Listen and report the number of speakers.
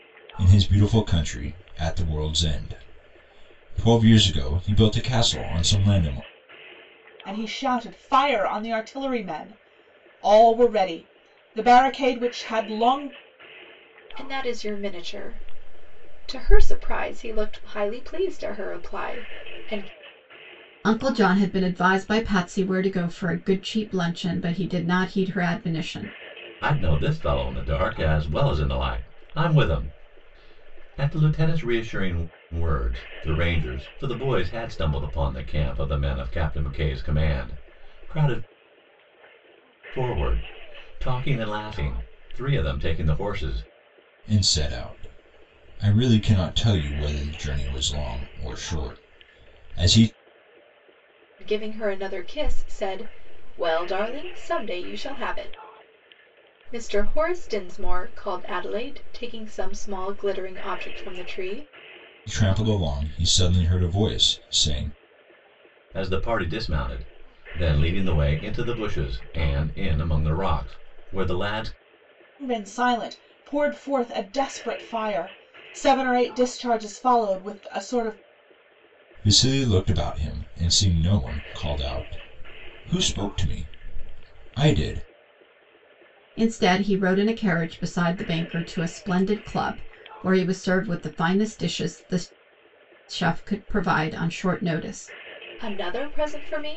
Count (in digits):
5